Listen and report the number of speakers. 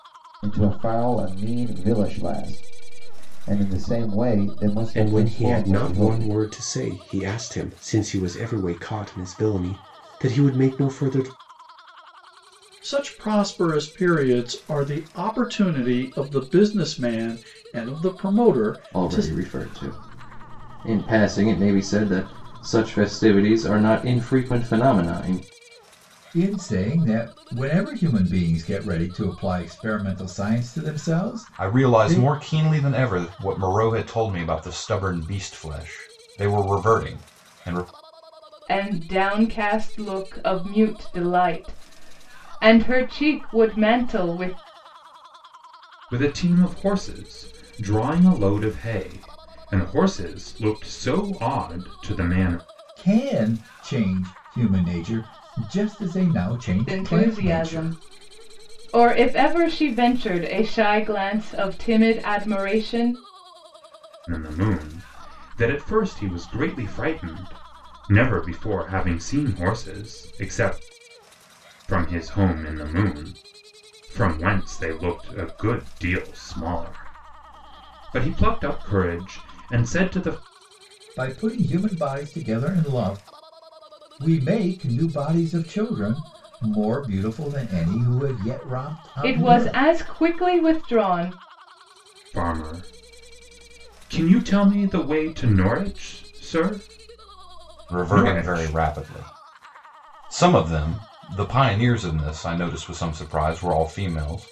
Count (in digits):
8